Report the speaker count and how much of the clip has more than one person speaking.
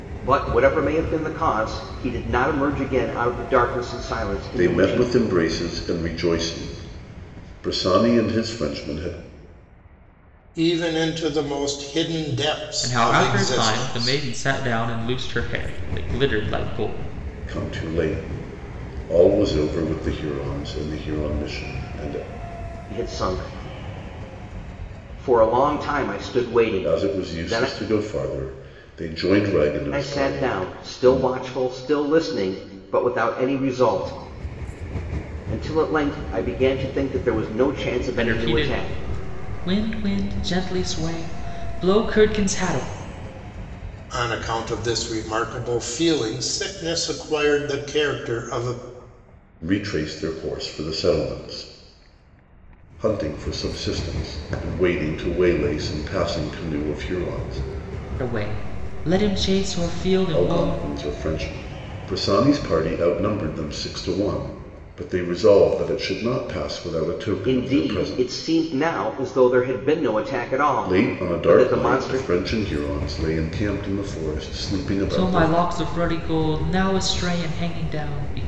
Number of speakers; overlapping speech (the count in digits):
4, about 11%